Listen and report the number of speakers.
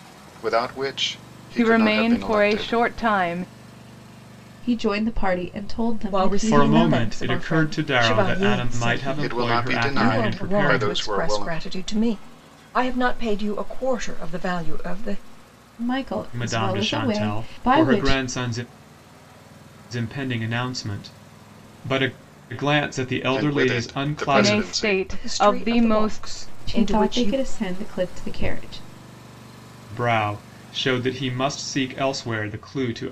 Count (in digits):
5